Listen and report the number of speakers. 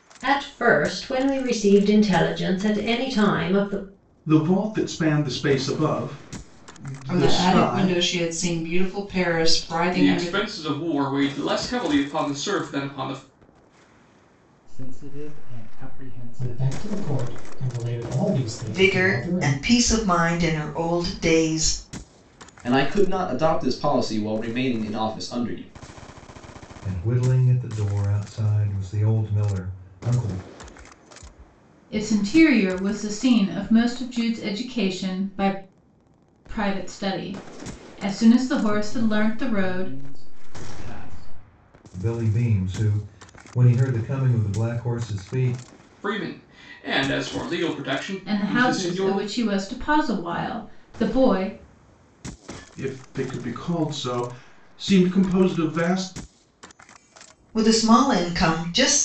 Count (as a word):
ten